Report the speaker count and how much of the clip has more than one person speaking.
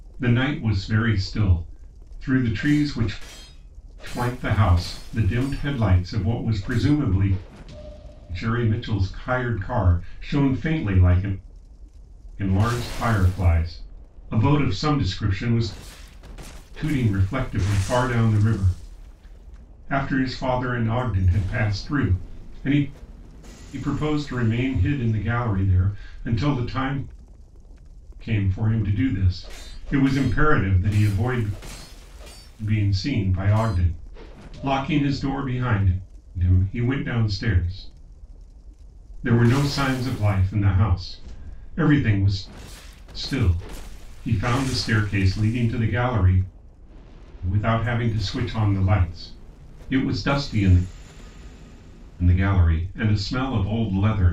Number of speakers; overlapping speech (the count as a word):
one, no overlap